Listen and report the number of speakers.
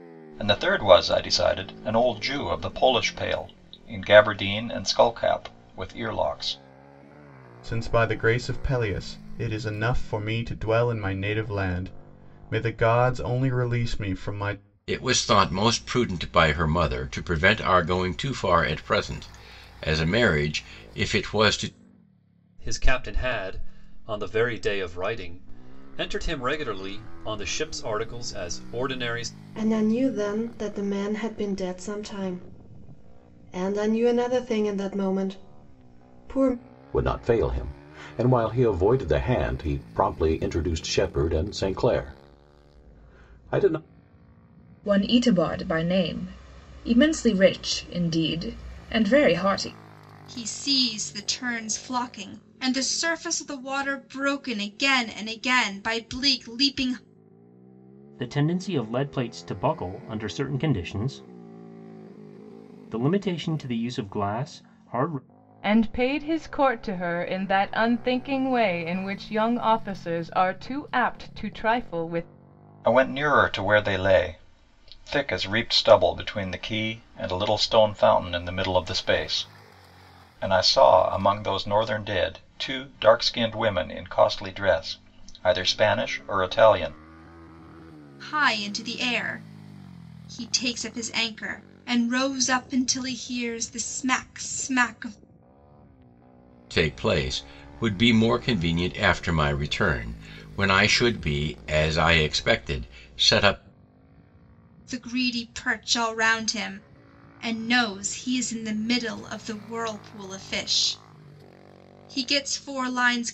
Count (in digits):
10